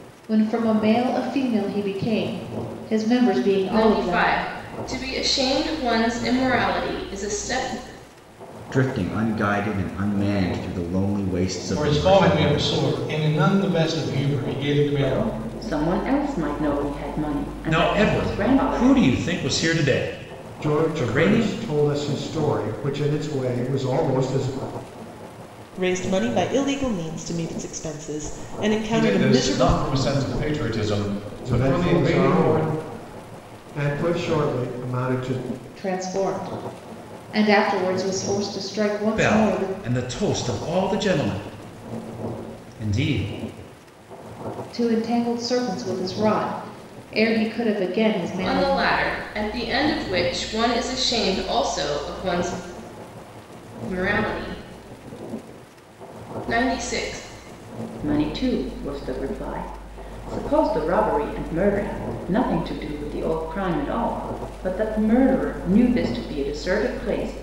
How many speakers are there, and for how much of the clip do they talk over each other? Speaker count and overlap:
nine, about 12%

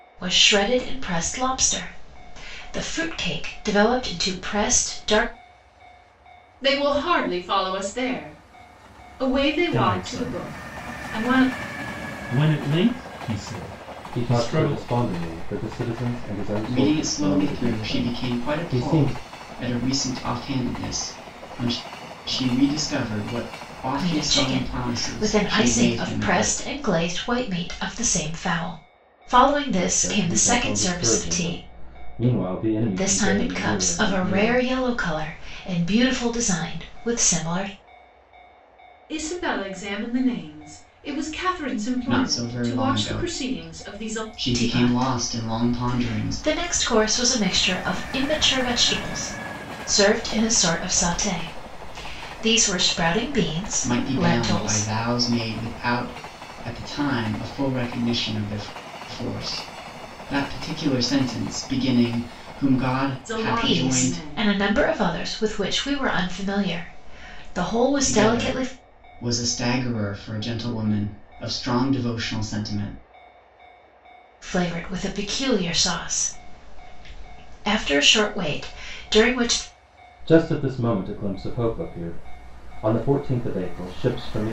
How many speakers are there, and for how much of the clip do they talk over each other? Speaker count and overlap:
five, about 22%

